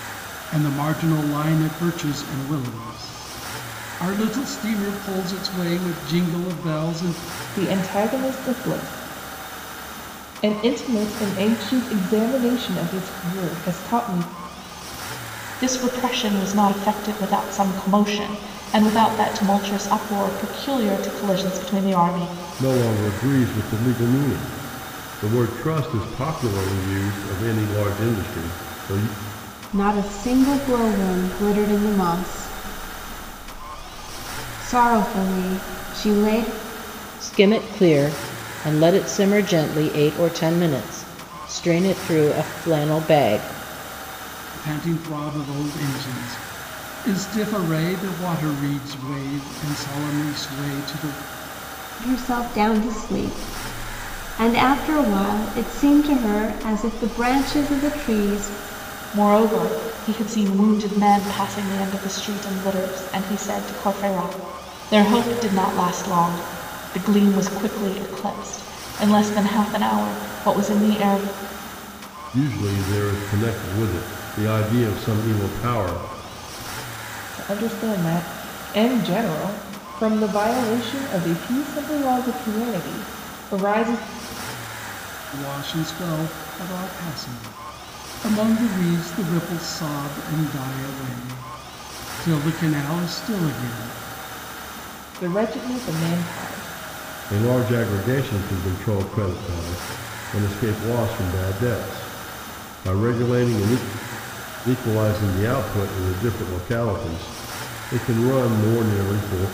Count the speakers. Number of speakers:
six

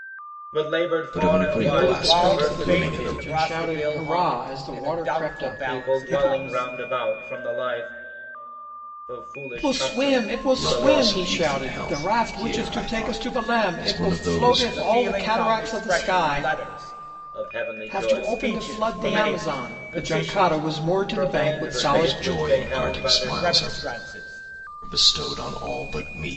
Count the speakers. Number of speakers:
four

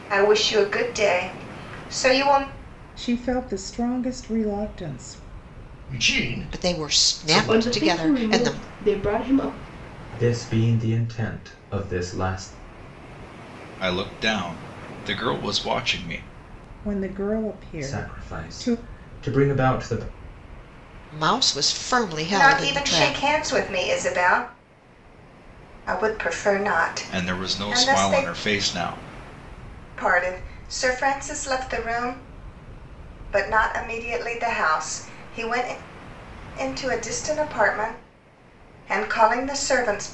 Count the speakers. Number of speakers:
seven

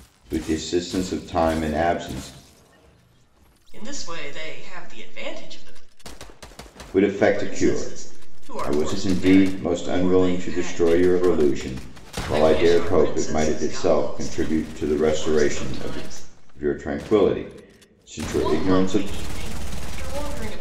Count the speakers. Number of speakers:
two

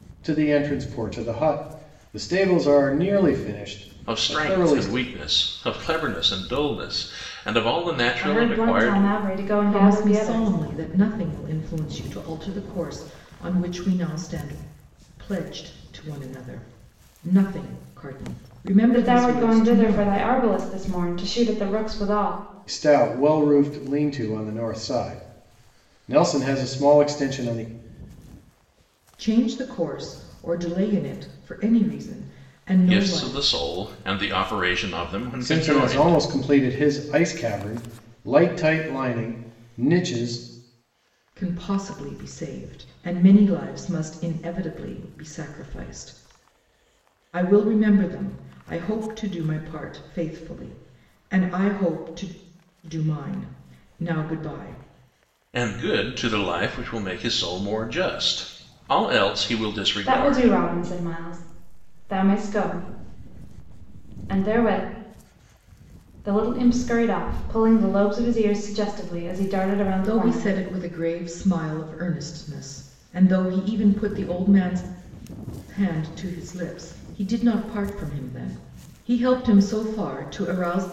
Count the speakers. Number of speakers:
four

